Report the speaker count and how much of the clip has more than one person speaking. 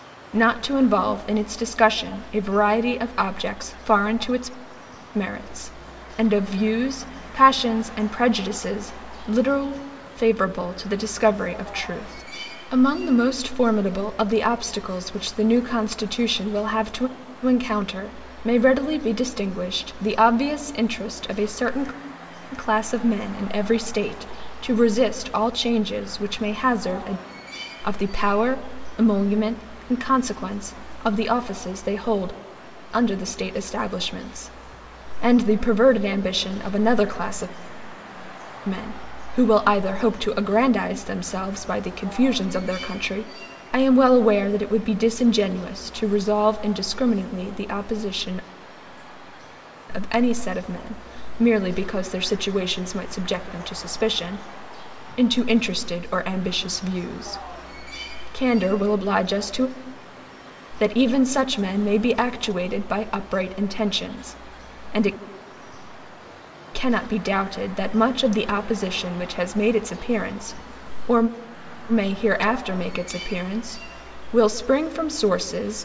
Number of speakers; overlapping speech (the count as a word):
one, no overlap